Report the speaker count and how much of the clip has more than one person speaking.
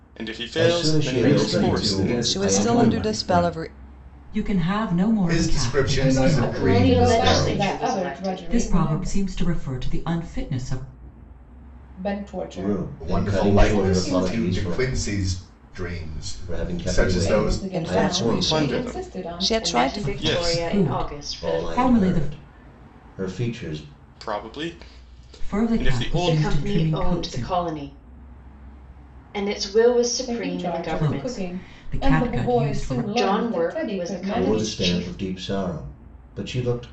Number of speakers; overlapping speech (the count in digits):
9, about 59%